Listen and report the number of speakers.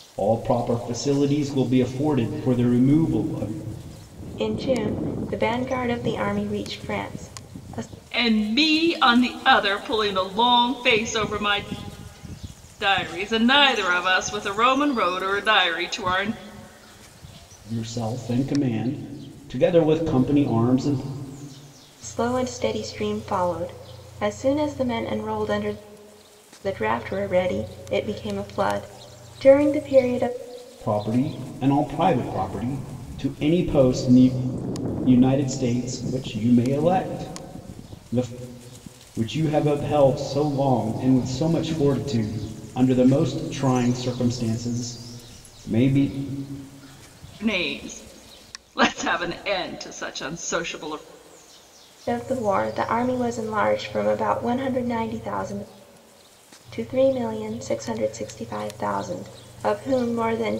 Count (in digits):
3